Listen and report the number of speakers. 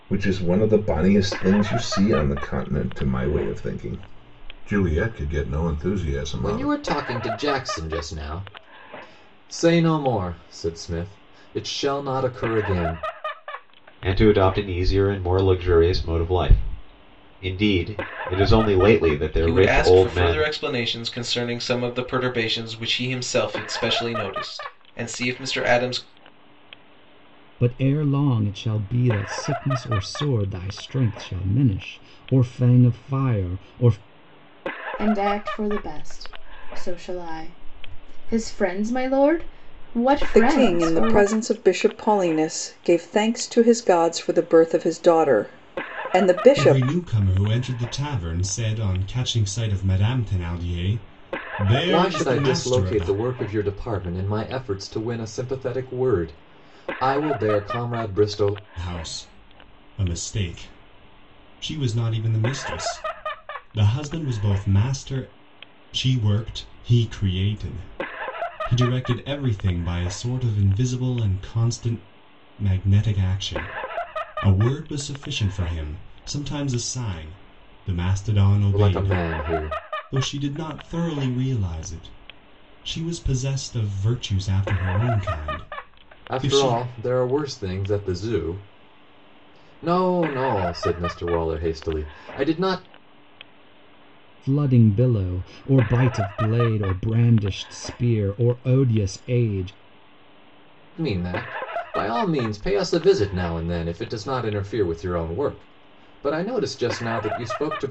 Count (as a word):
eight